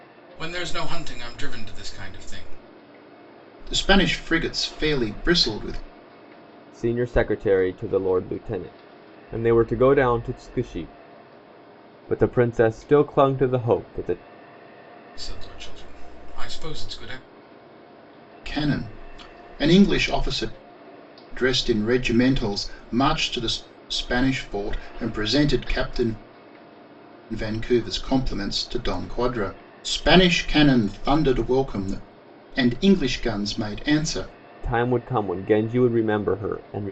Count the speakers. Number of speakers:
3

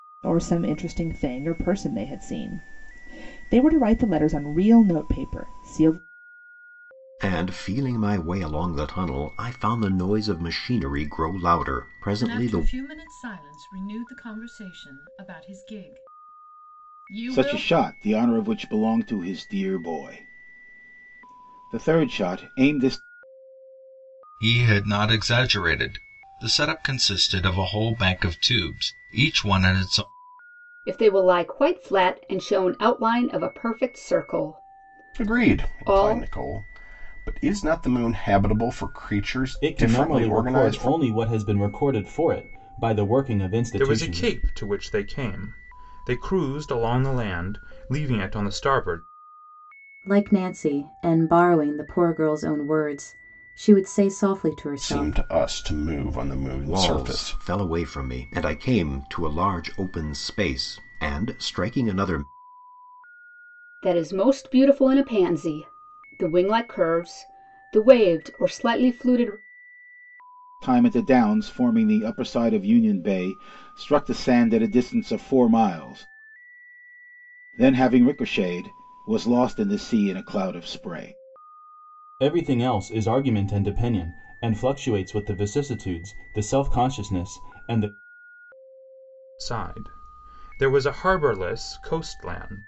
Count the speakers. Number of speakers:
10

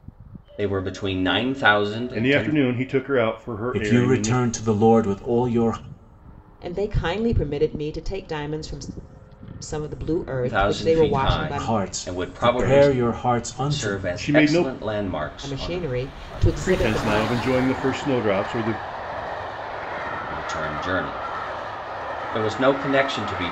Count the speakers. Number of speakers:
4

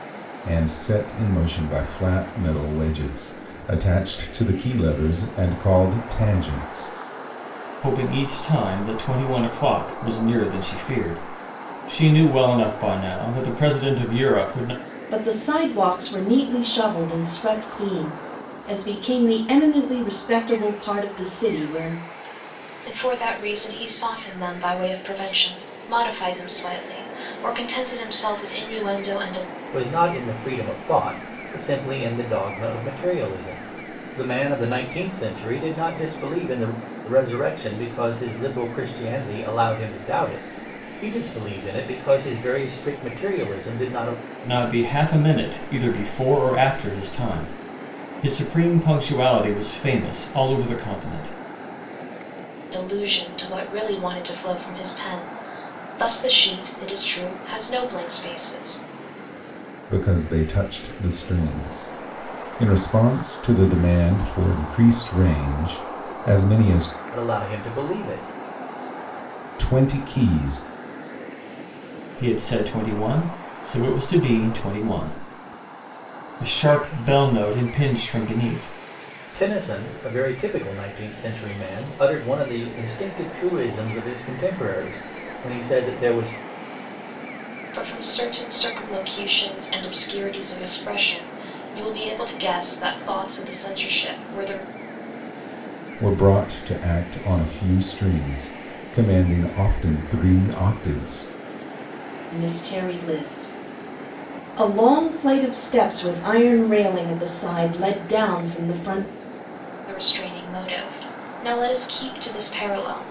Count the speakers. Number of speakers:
5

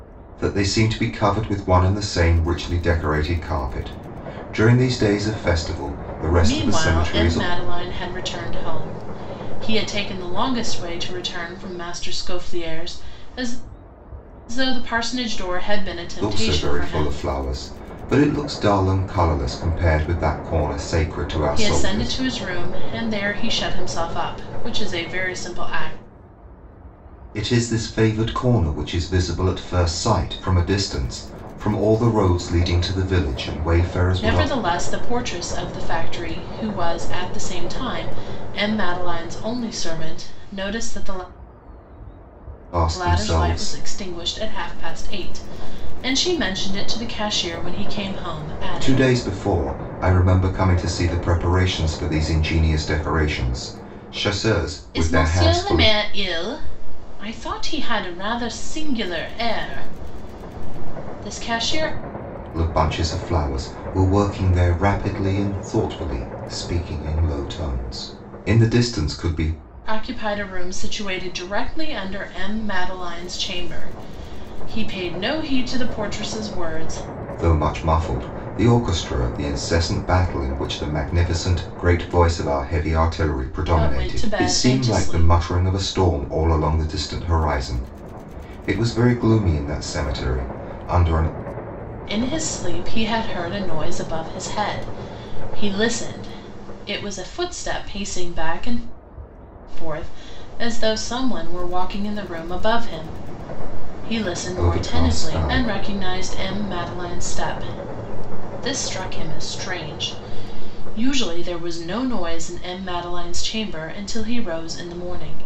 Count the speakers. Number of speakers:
2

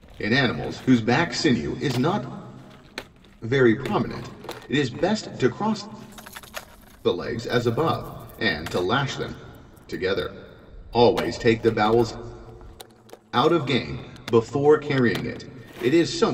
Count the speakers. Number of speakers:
1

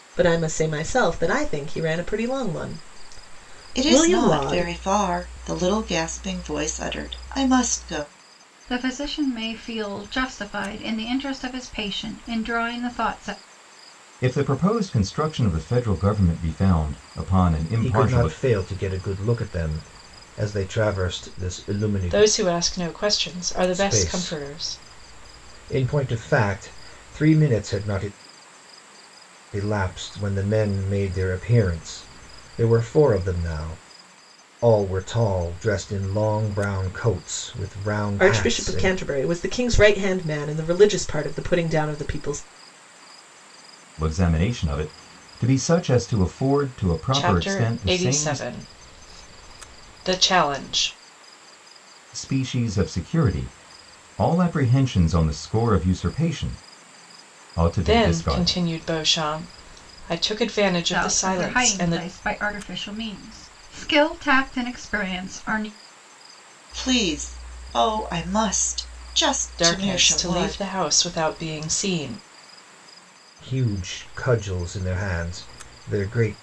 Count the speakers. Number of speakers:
6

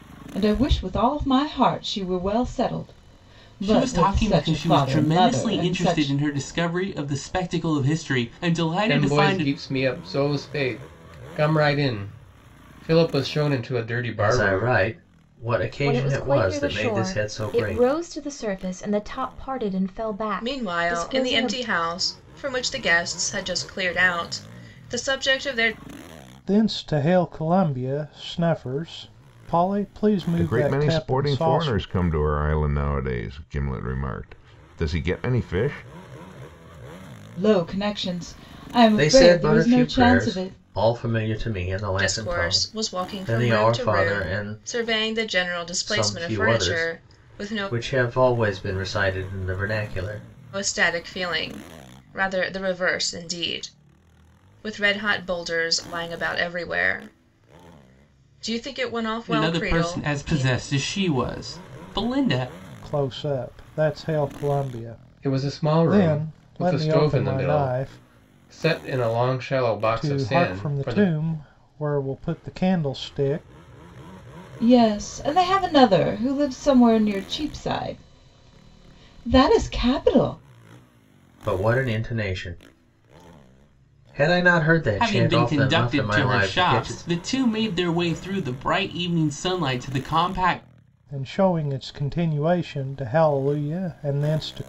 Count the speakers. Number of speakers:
8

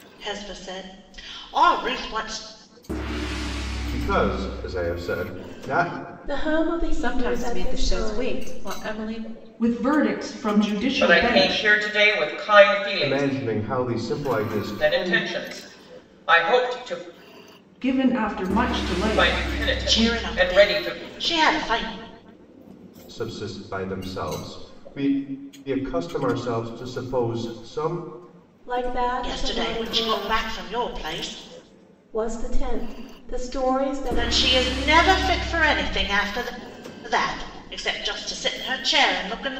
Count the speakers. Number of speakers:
6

